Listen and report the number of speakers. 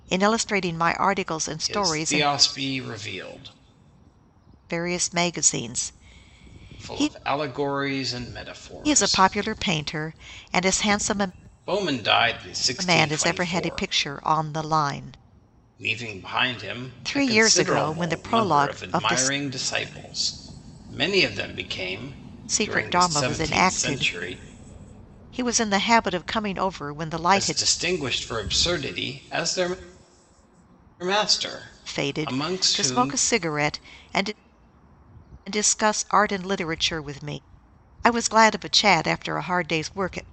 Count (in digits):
2